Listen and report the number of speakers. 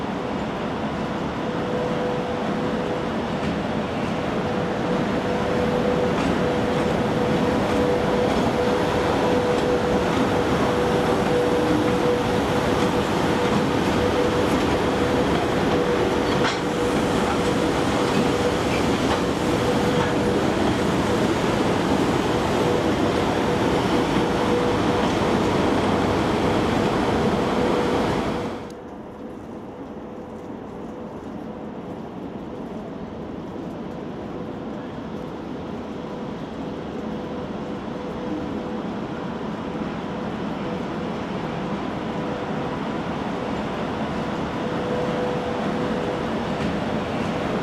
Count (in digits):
0